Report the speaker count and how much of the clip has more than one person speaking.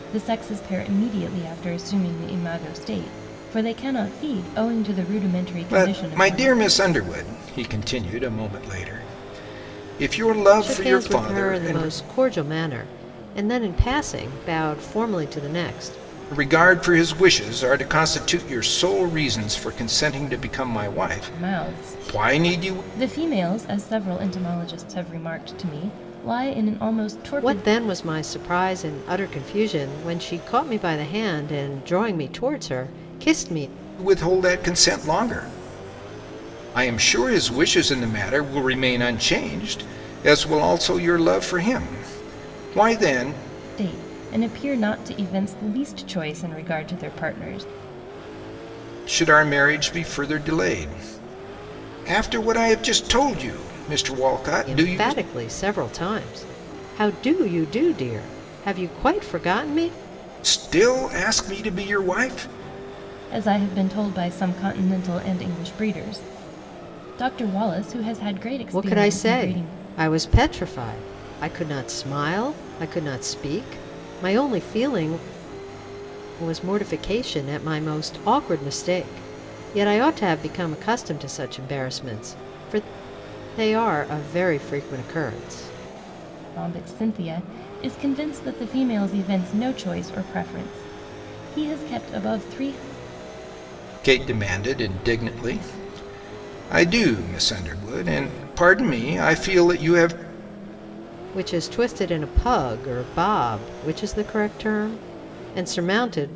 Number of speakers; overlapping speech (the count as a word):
three, about 5%